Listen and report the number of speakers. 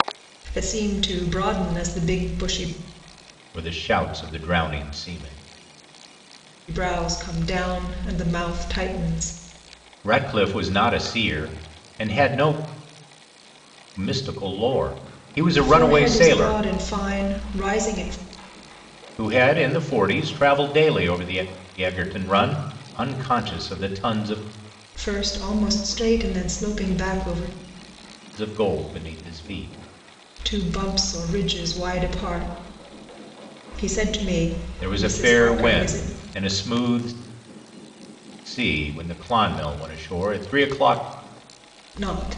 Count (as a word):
two